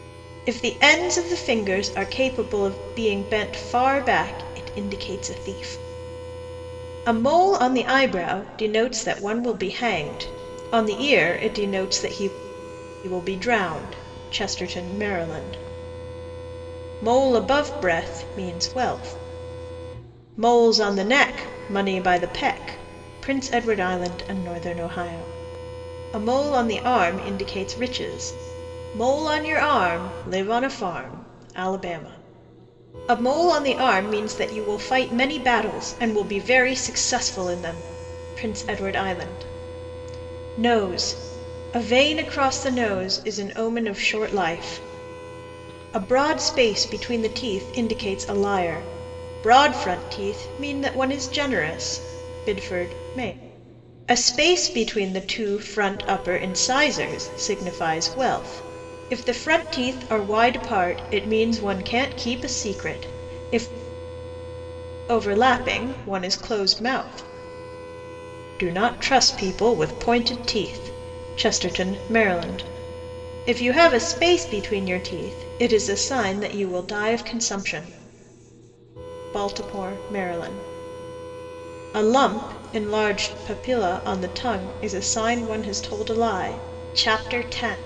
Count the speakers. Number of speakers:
one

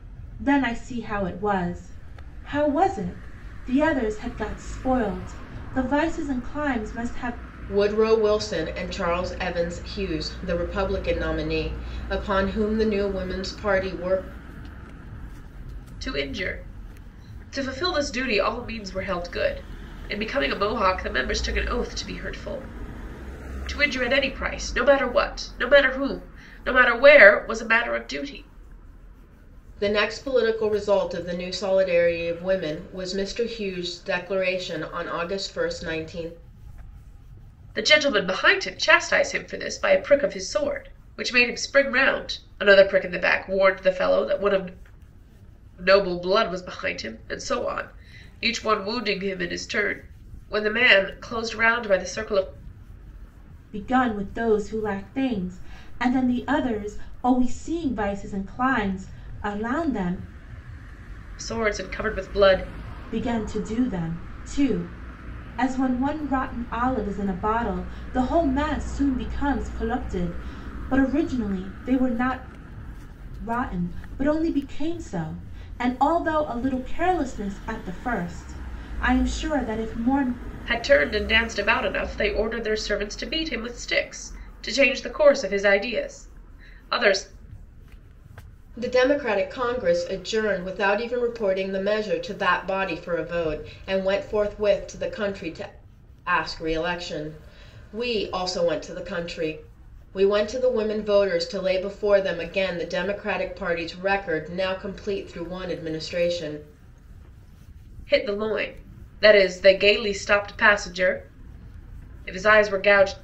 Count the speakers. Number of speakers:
three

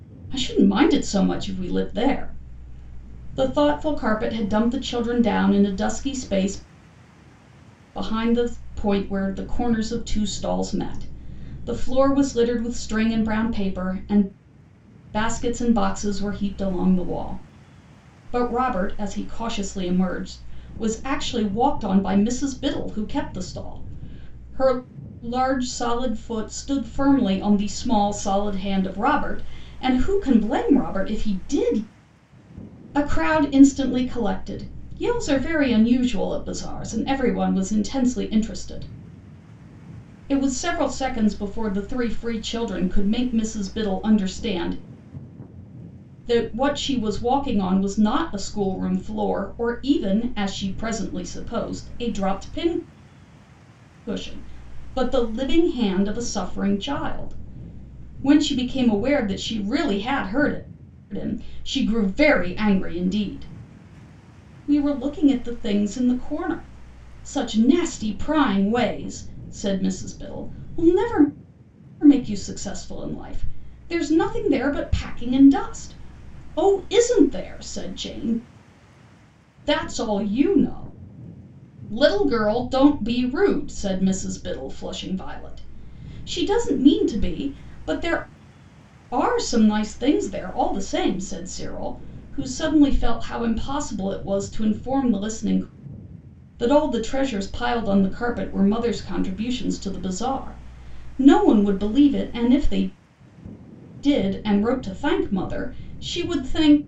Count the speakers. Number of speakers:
one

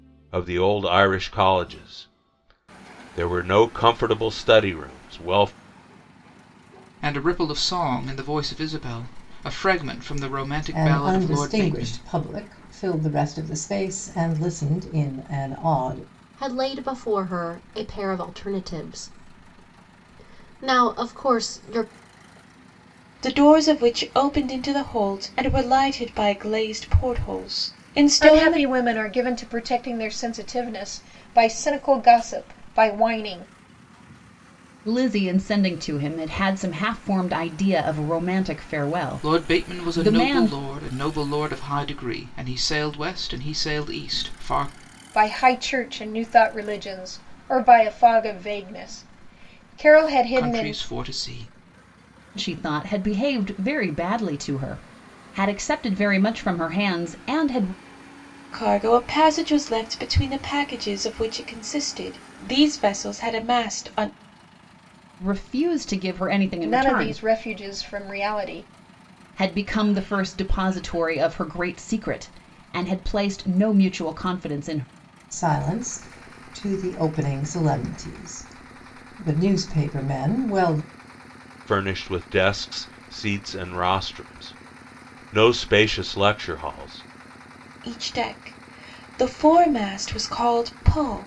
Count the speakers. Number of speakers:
seven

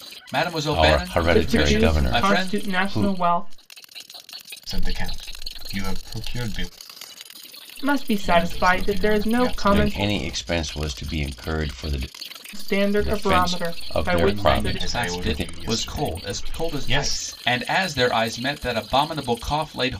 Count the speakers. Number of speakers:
four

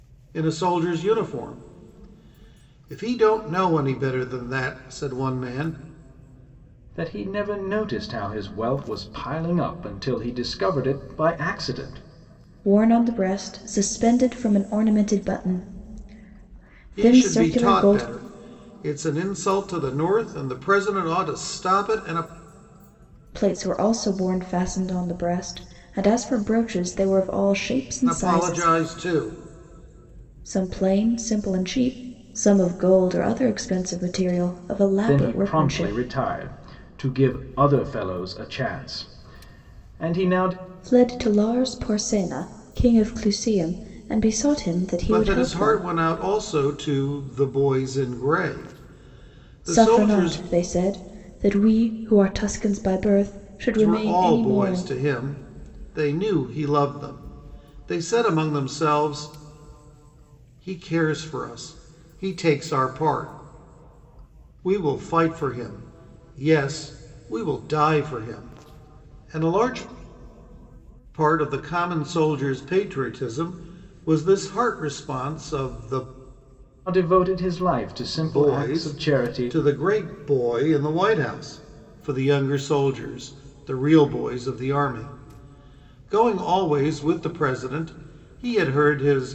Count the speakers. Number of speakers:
three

